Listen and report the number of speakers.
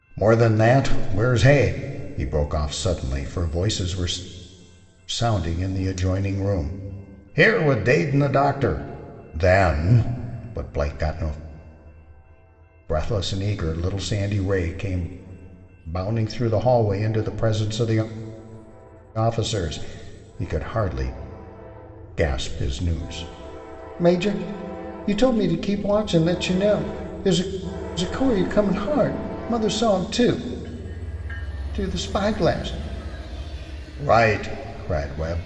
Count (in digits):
1